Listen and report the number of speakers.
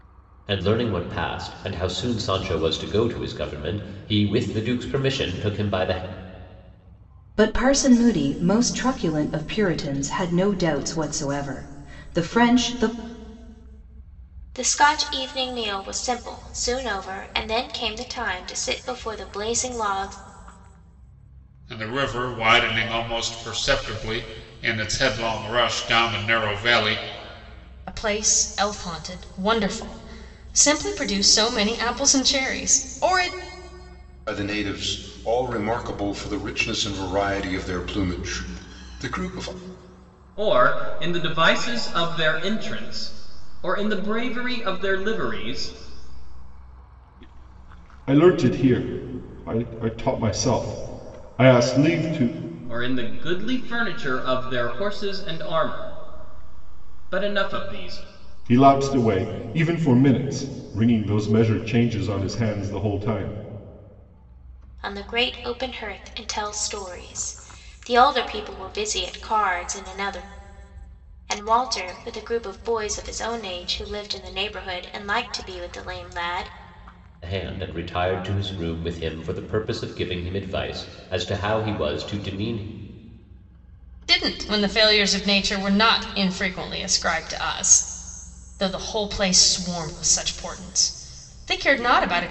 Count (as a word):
eight